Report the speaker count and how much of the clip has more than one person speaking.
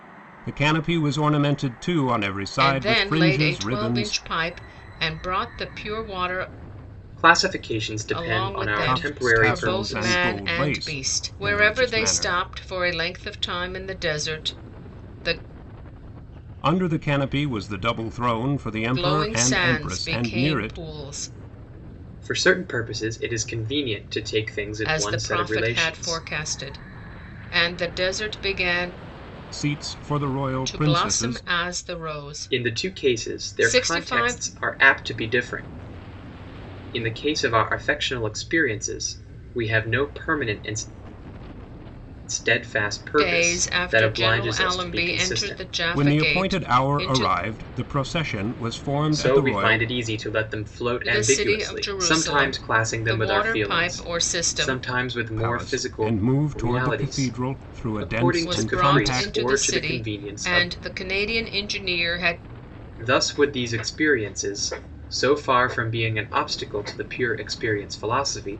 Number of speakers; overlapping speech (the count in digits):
3, about 37%